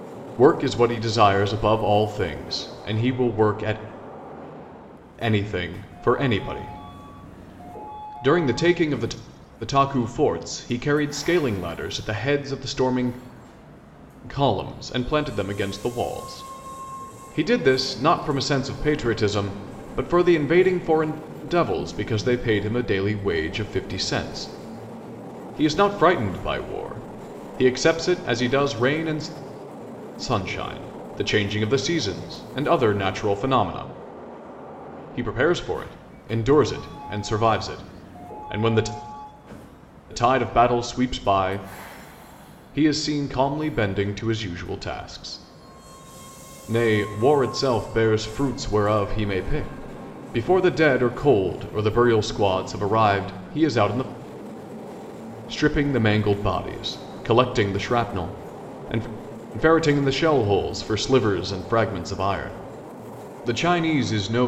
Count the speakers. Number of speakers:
1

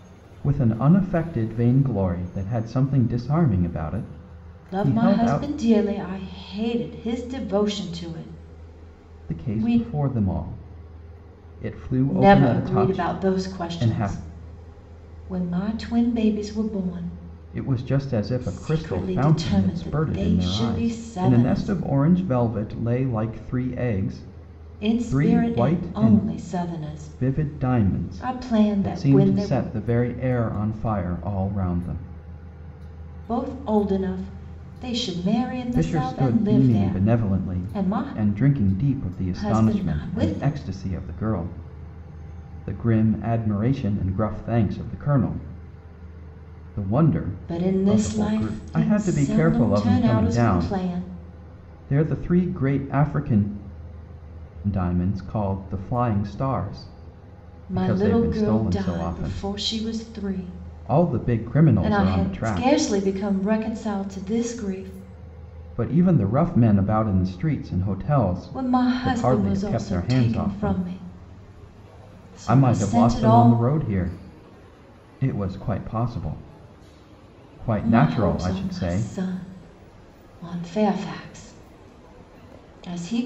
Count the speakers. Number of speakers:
2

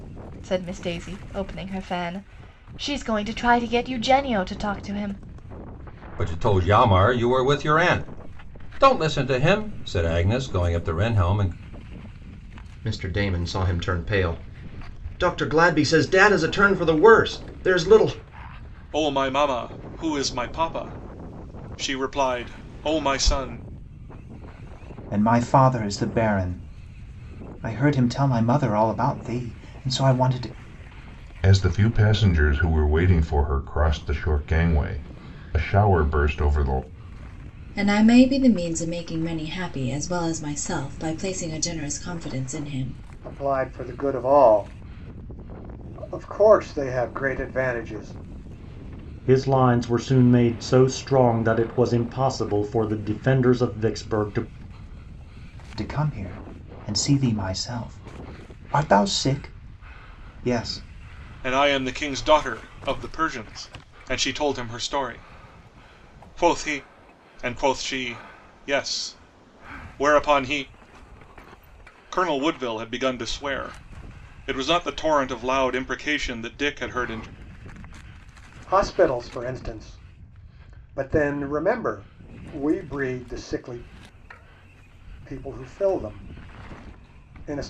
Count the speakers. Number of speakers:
9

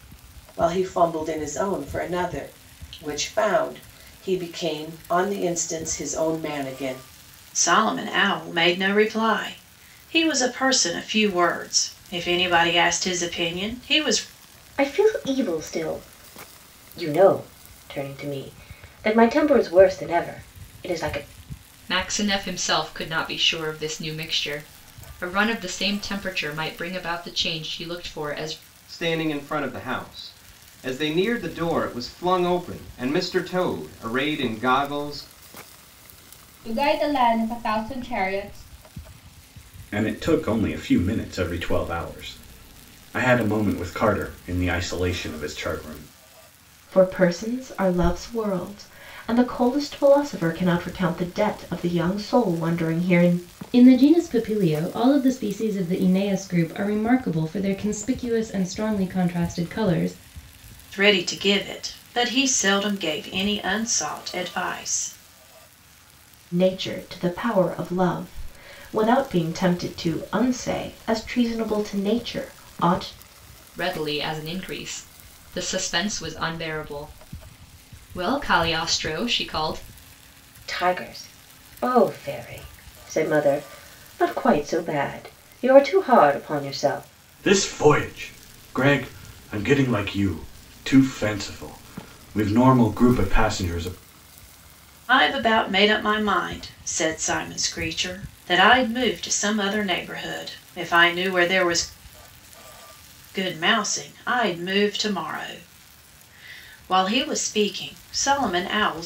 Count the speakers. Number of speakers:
9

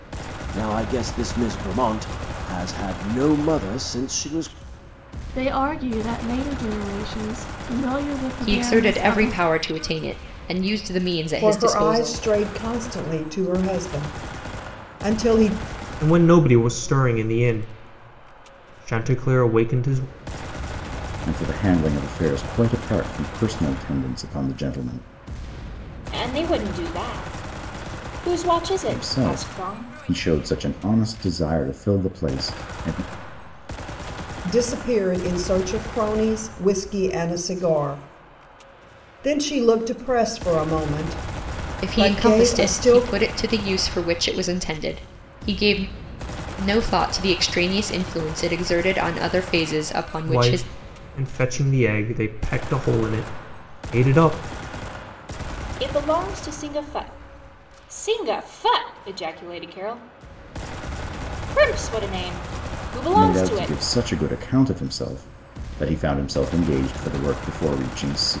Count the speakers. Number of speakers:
7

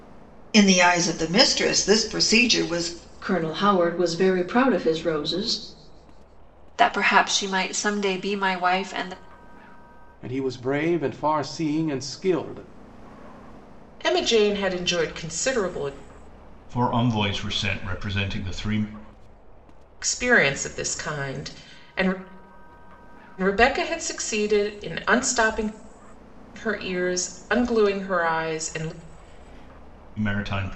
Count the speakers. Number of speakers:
6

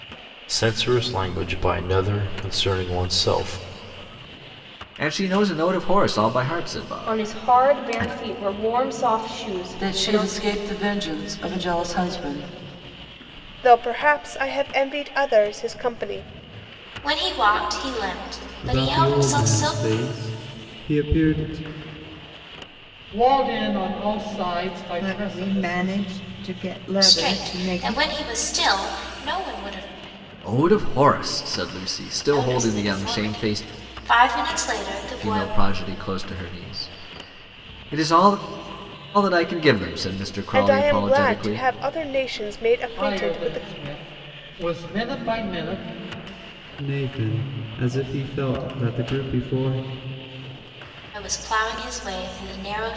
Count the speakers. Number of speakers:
9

